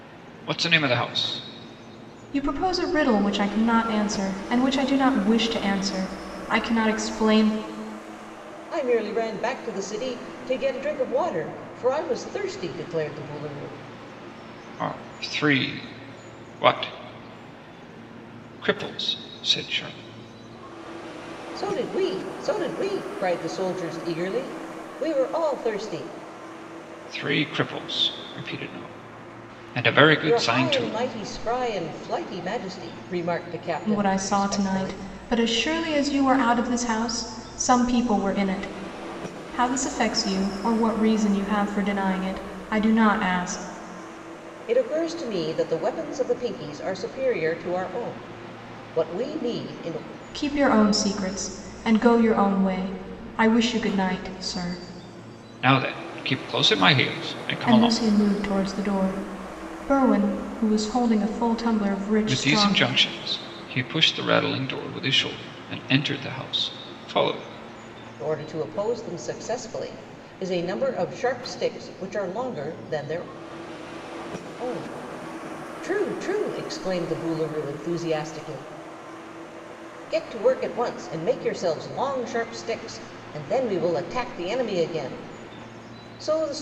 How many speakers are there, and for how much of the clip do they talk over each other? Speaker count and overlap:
three, about 4%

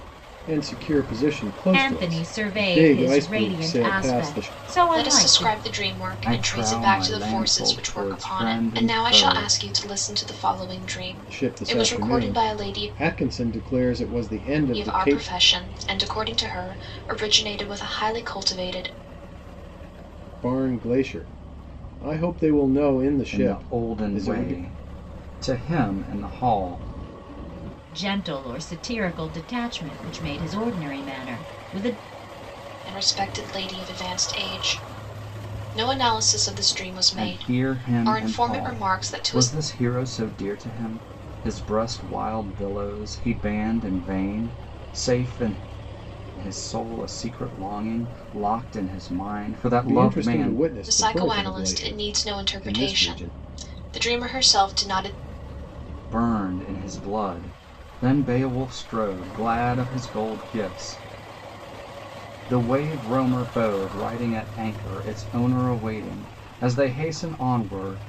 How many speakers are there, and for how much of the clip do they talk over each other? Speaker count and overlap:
four, about 23%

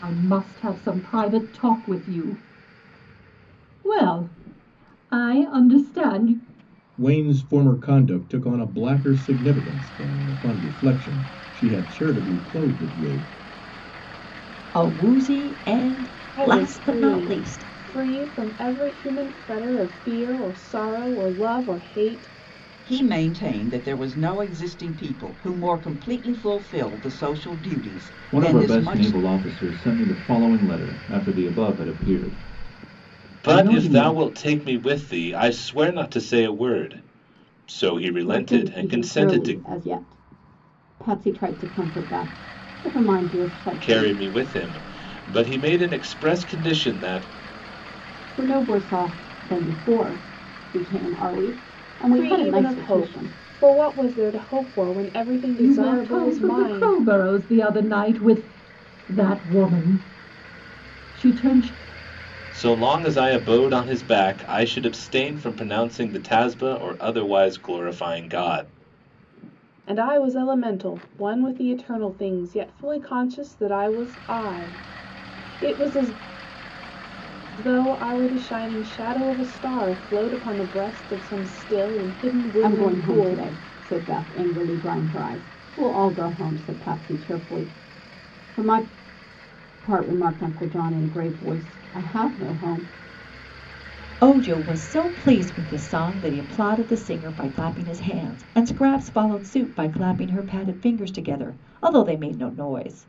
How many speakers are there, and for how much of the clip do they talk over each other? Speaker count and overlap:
eight, about 8%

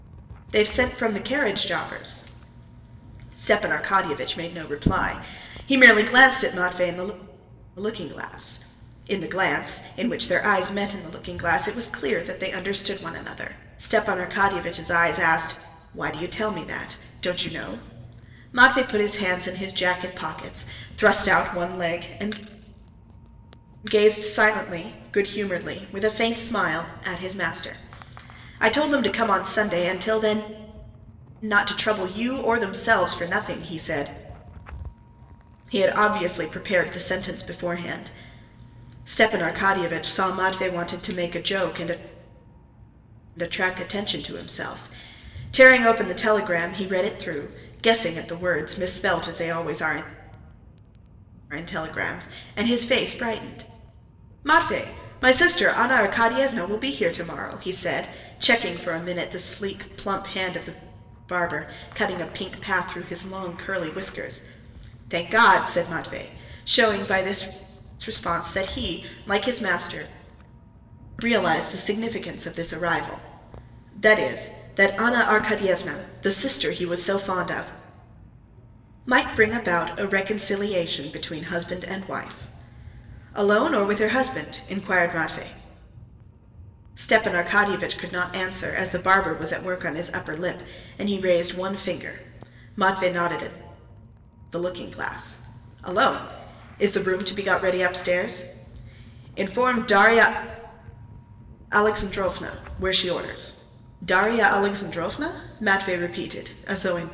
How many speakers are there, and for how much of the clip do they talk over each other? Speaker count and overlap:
one, no overlap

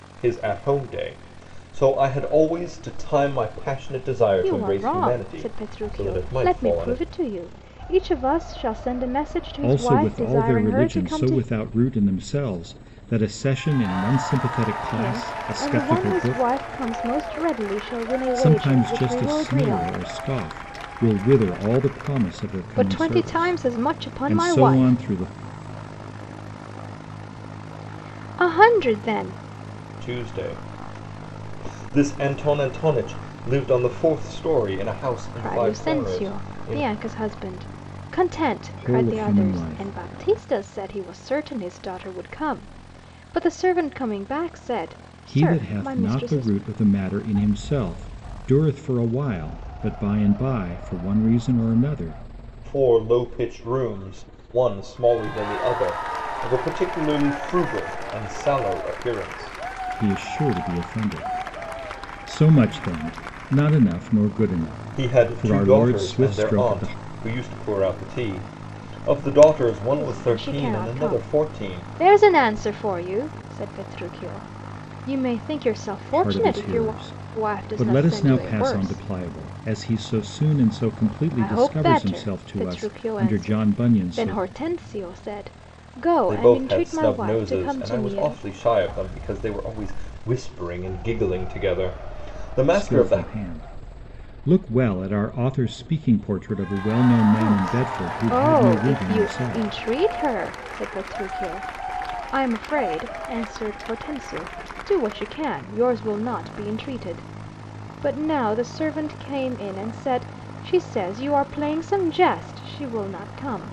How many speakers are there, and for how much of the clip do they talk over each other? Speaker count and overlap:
three, about 26%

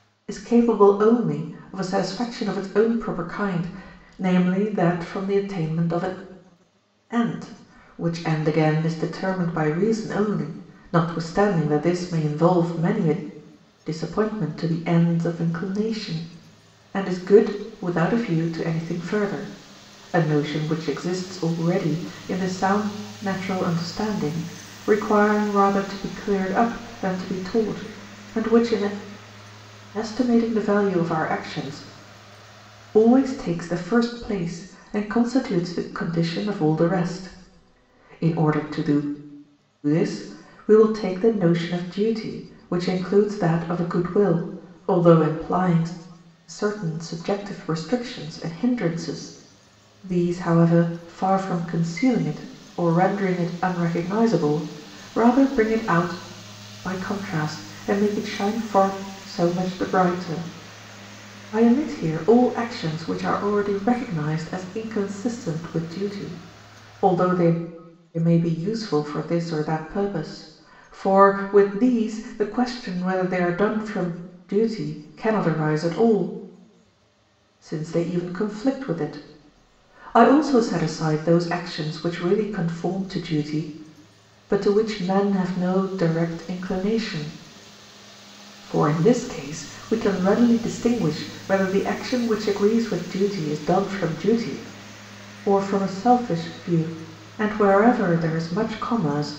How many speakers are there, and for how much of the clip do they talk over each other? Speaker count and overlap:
one, no overlap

